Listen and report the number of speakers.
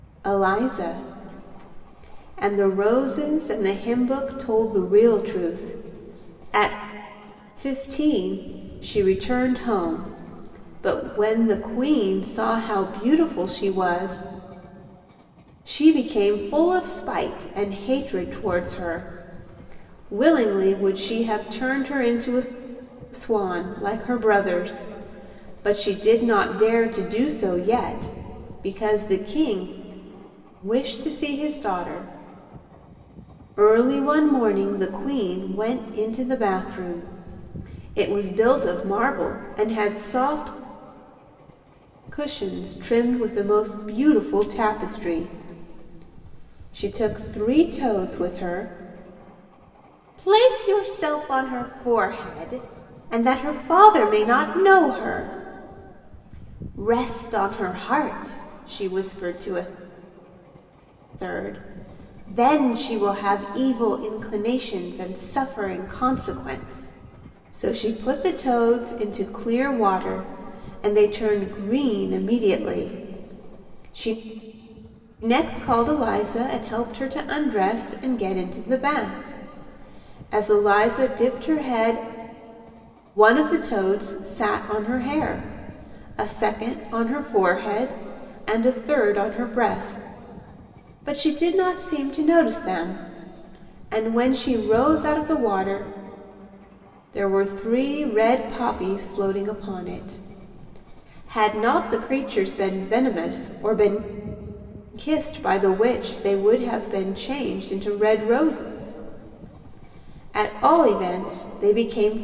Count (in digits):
1